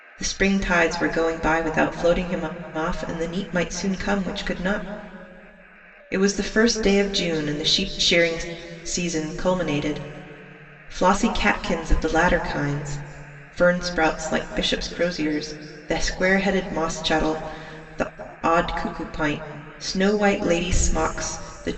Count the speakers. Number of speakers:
1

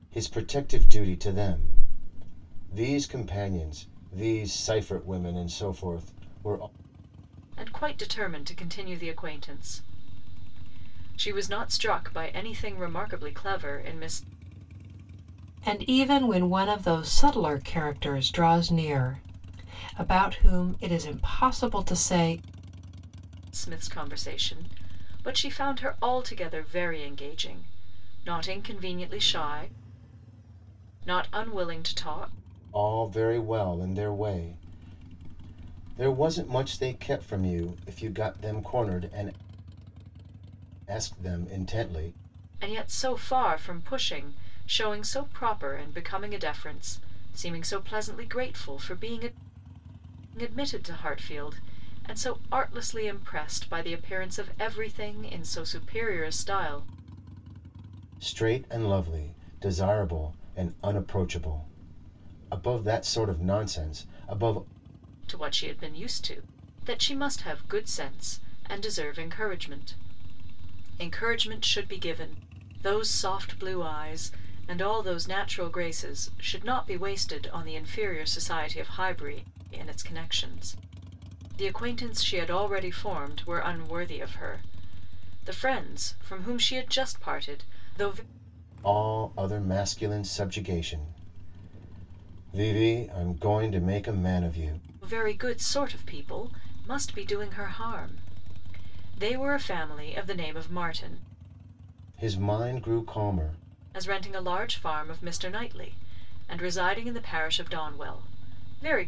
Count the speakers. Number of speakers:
3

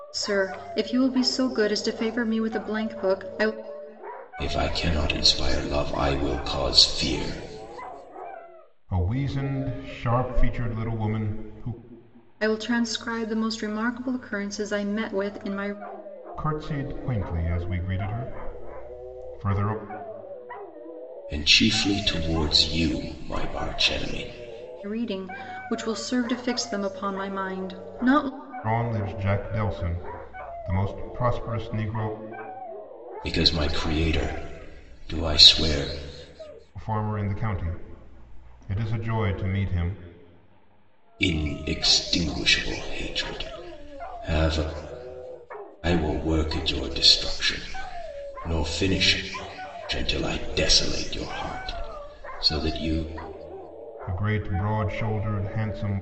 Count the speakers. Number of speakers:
3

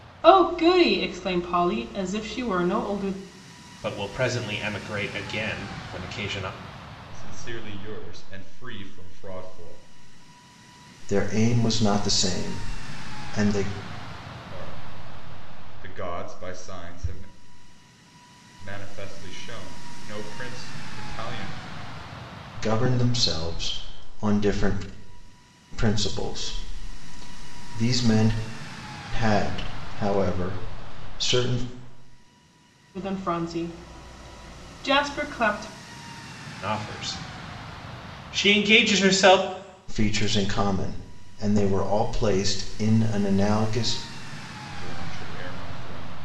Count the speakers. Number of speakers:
4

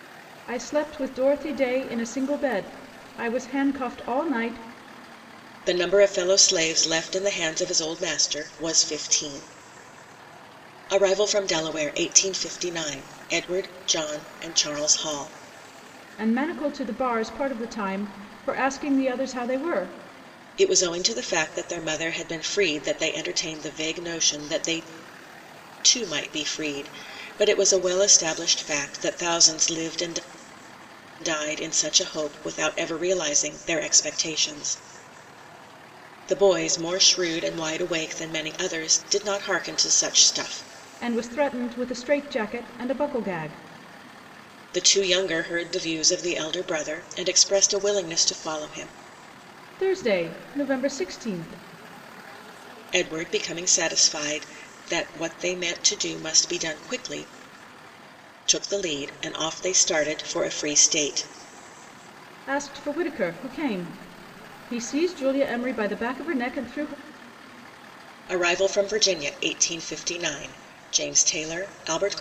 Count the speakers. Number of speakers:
2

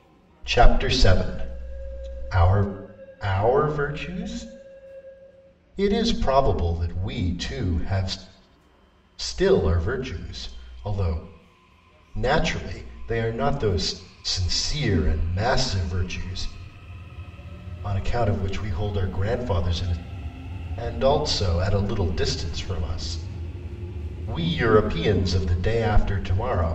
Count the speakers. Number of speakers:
1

